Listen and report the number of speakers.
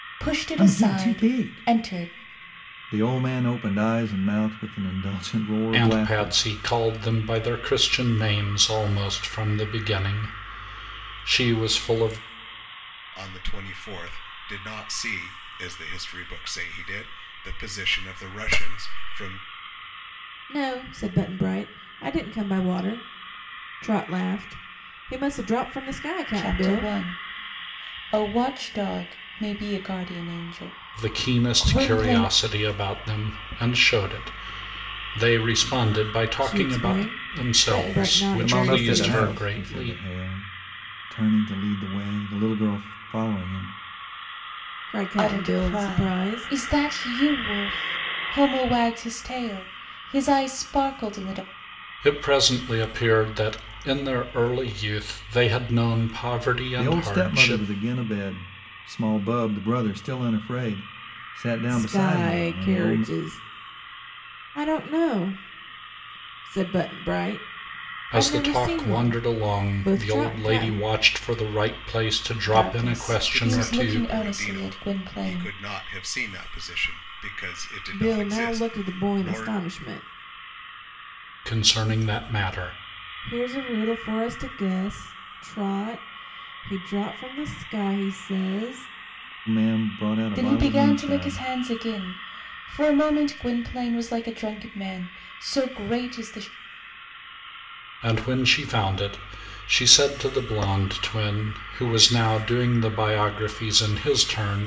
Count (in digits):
5